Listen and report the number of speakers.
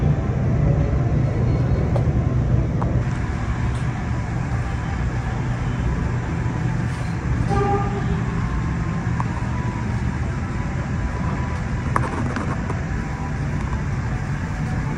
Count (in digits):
0